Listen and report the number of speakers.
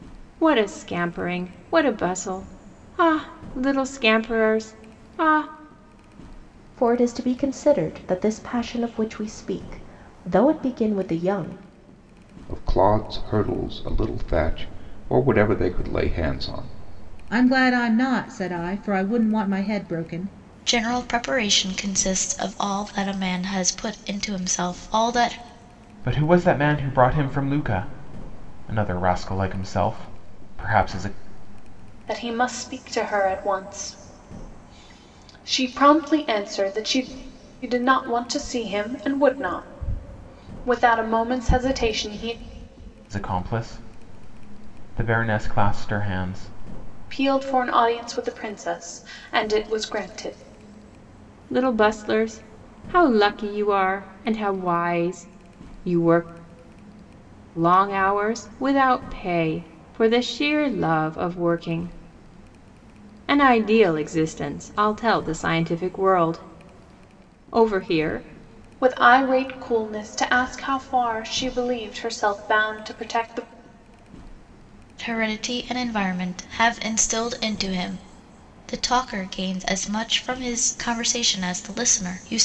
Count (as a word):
seven